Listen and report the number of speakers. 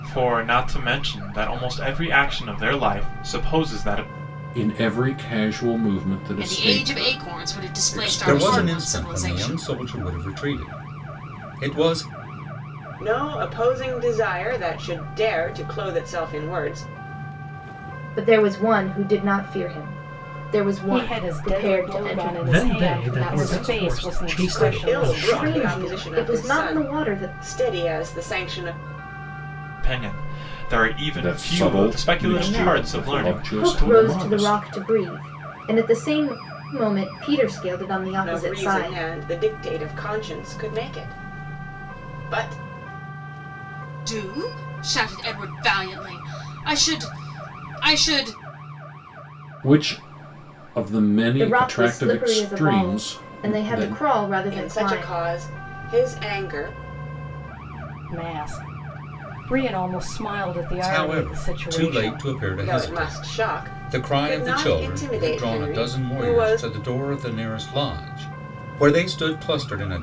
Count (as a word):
eight